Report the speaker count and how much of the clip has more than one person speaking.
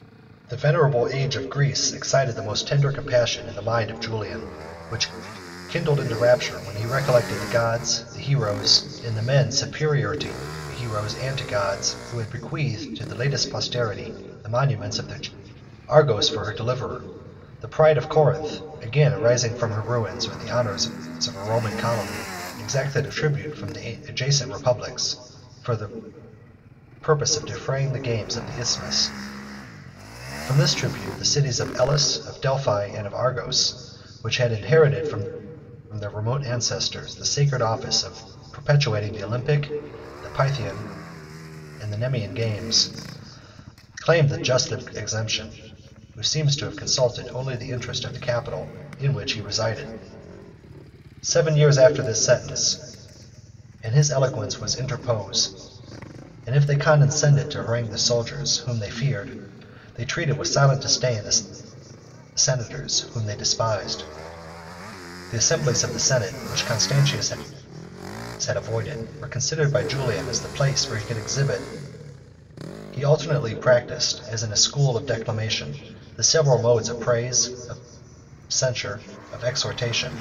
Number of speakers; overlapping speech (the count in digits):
1, no overlap